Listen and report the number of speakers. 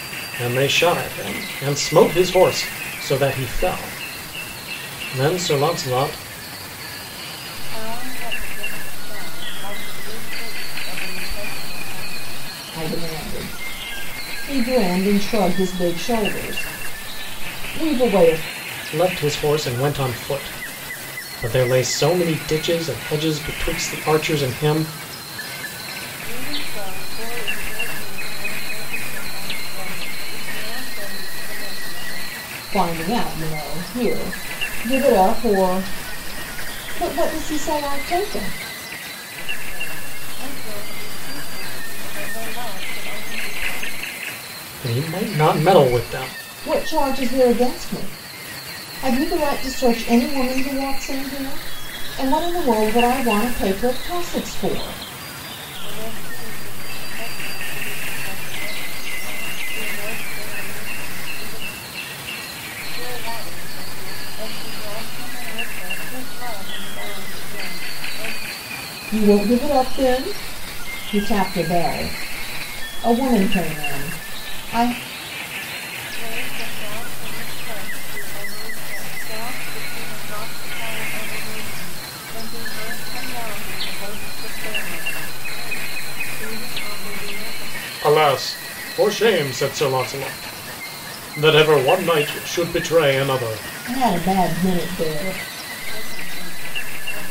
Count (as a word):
three